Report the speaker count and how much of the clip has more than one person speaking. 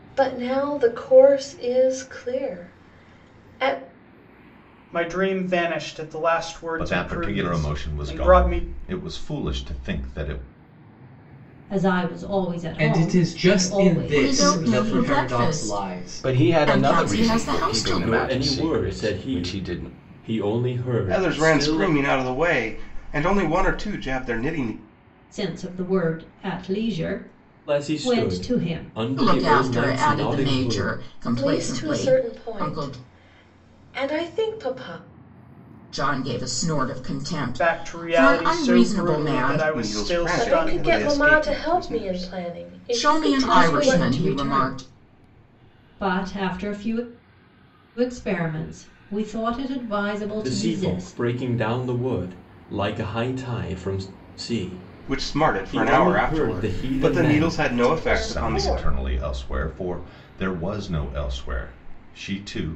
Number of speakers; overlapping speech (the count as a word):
nine, about 41%